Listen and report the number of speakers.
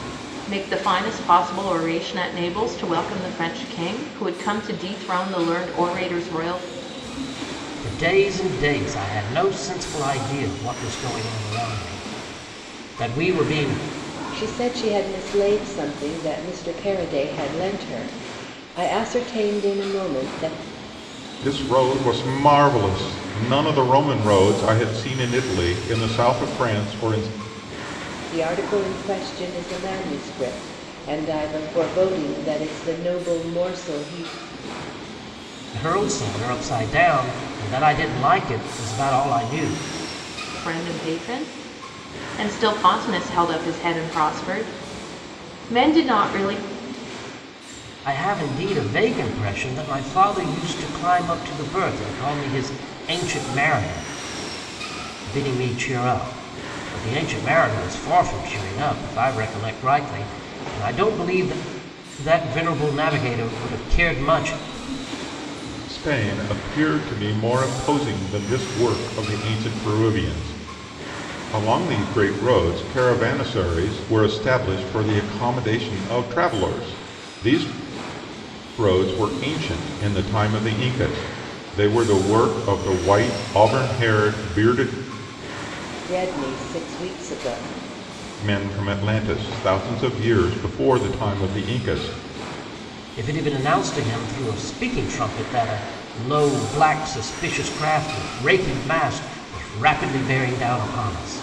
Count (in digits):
4